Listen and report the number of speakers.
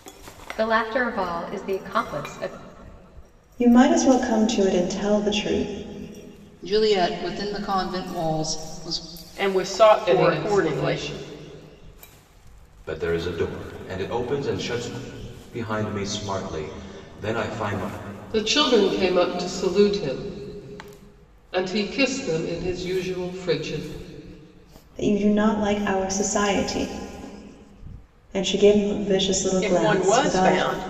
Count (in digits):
6